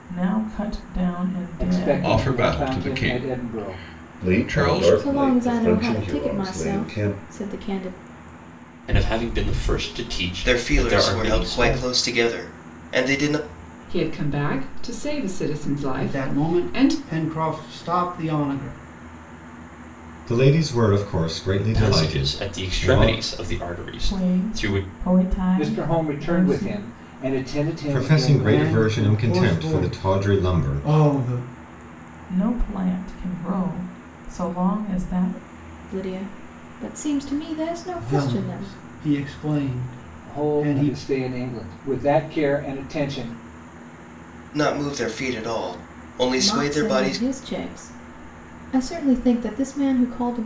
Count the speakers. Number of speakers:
ten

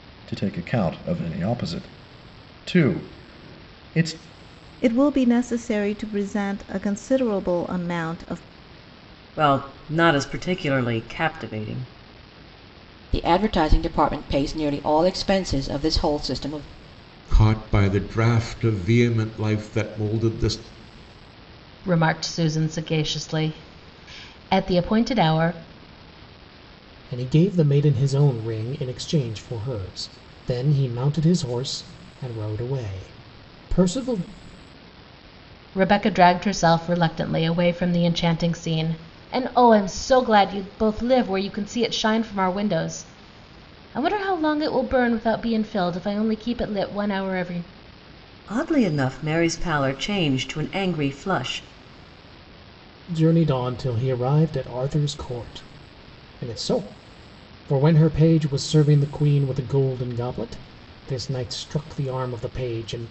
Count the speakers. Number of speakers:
seven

